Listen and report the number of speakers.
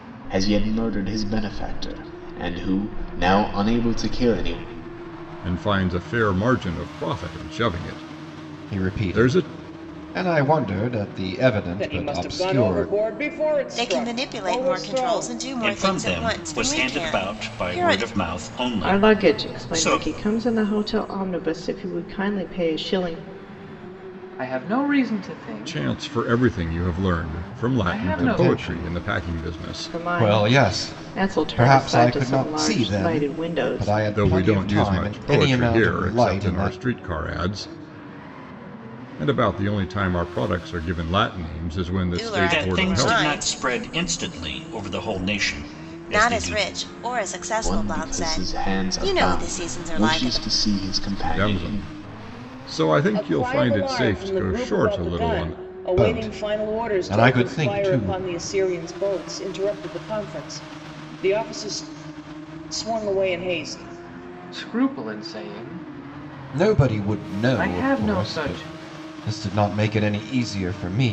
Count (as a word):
eight